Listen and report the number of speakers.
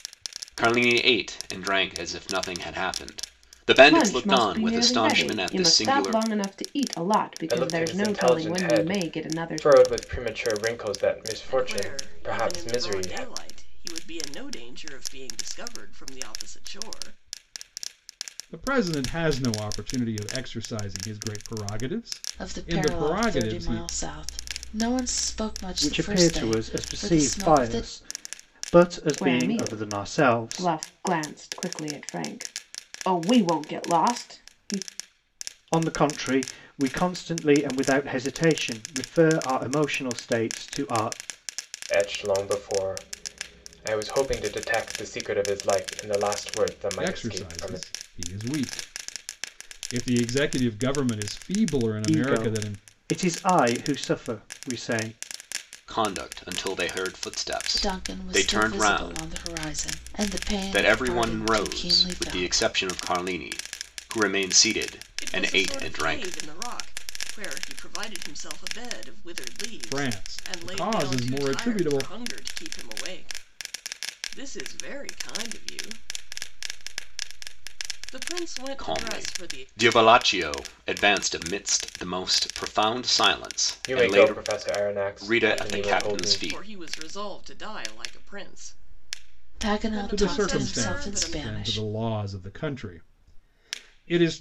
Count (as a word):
seven